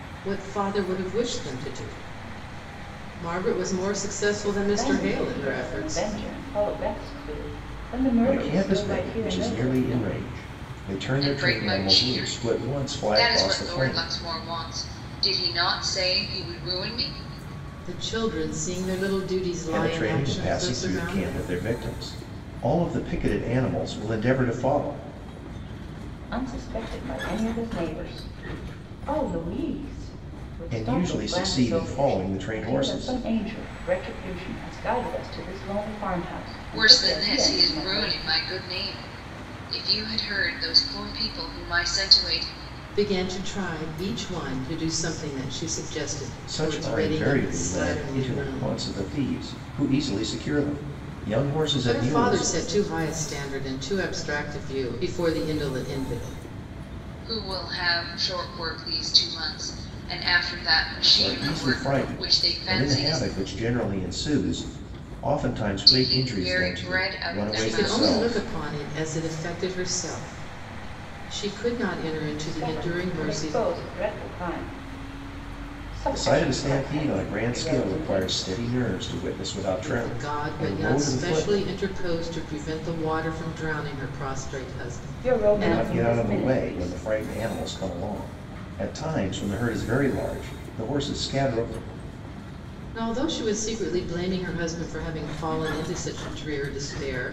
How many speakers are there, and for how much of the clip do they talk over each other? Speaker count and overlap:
4, about 28%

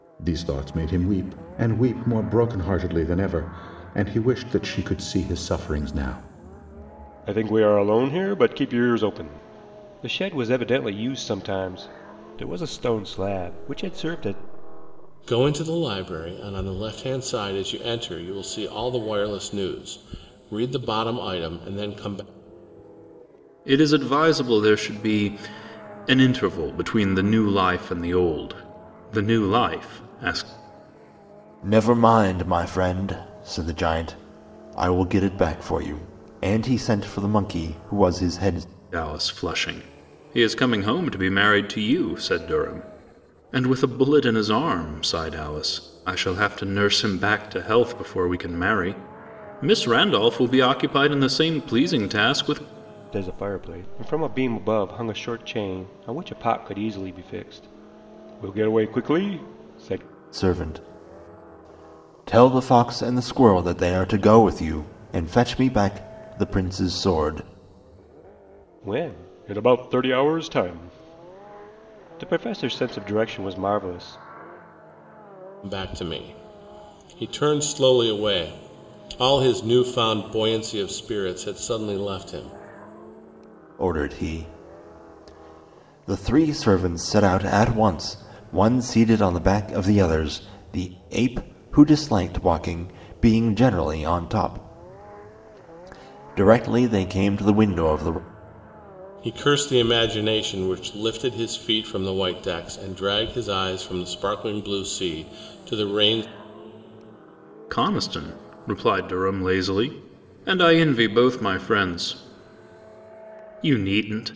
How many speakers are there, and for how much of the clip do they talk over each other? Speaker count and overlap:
5, no overlap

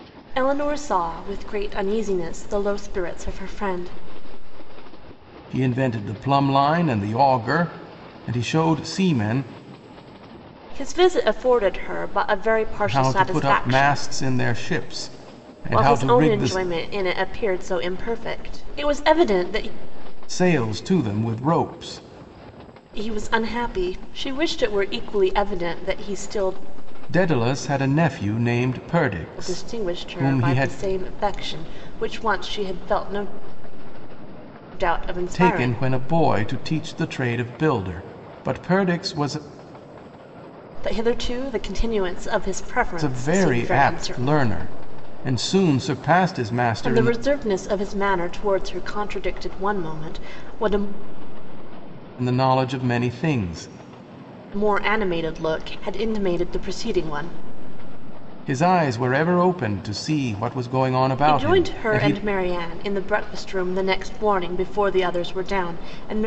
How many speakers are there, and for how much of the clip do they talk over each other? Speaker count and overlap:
2, about 10%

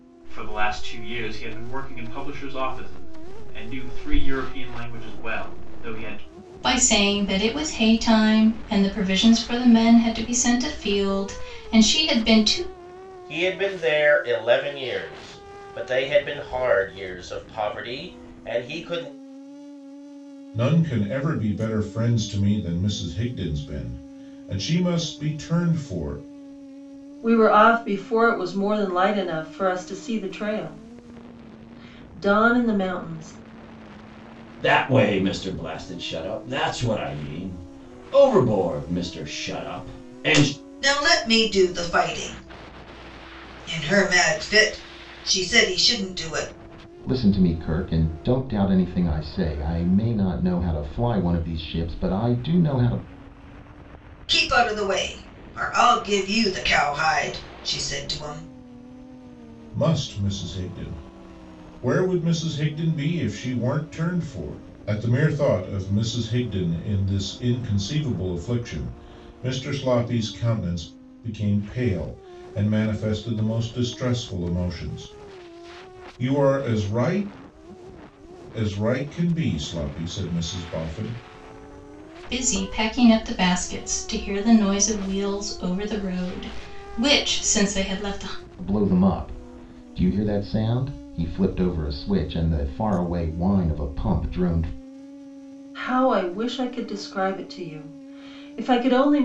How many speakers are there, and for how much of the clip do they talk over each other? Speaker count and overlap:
8, no overlap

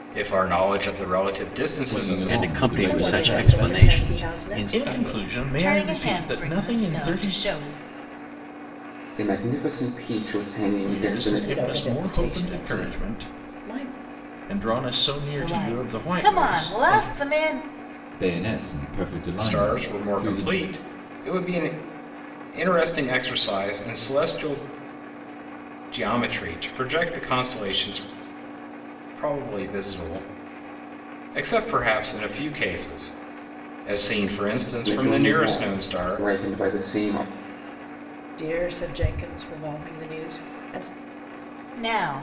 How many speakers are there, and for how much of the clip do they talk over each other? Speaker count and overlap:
7, about 29%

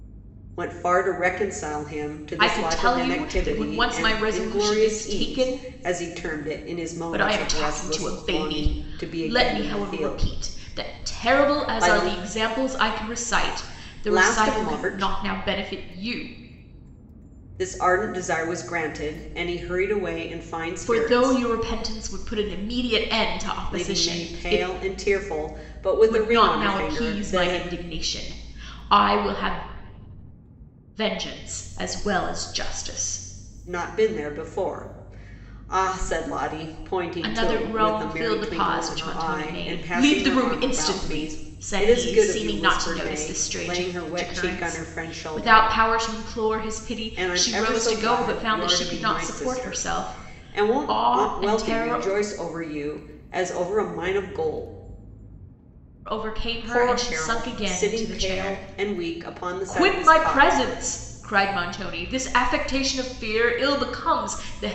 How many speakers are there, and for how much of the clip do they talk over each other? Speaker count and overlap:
2, about 43%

